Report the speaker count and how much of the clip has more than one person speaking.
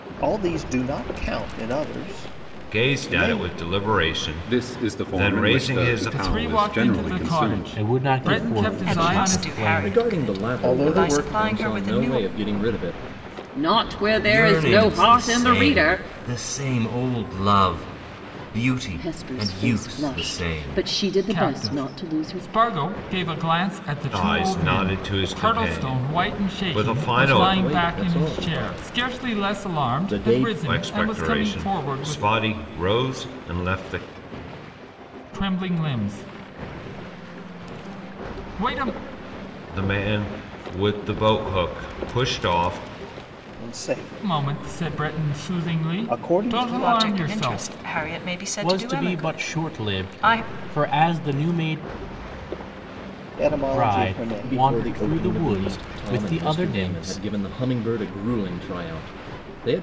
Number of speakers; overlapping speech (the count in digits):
10, about 51%